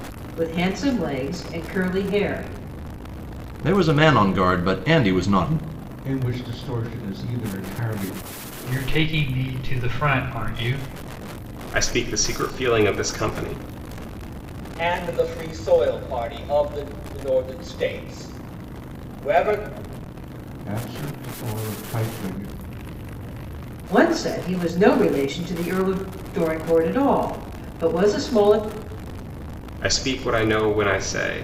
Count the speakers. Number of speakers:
six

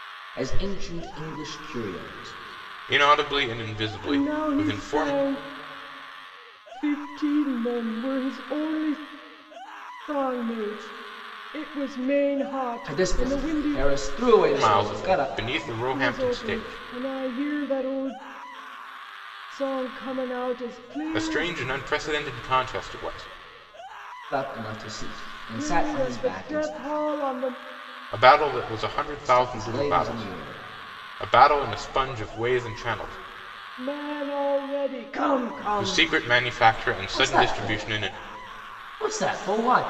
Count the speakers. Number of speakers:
three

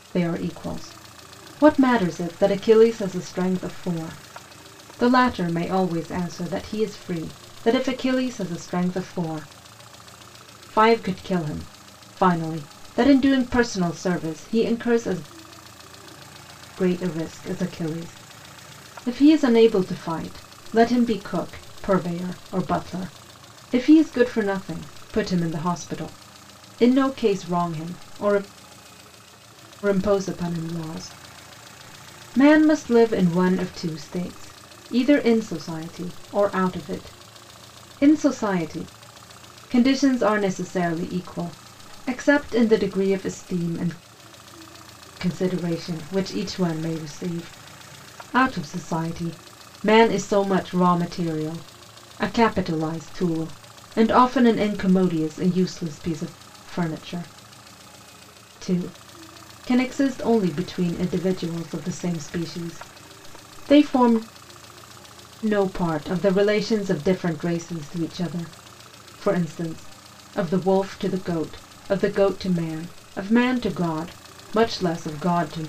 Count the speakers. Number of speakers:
one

